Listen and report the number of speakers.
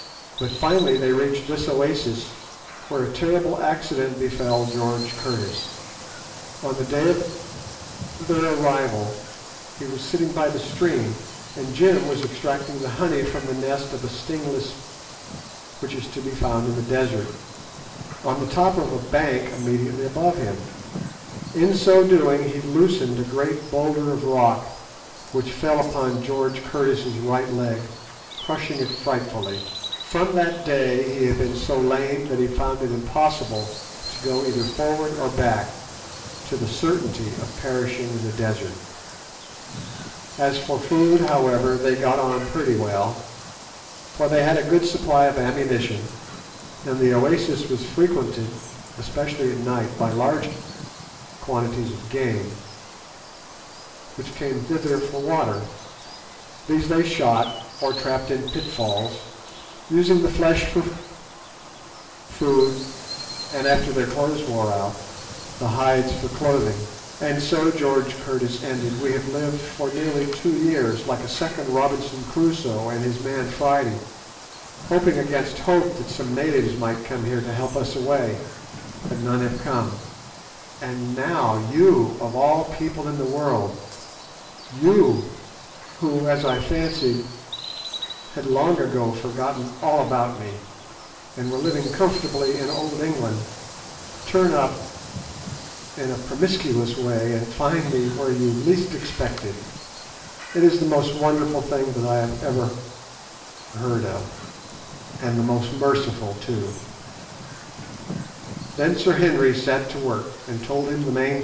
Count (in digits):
1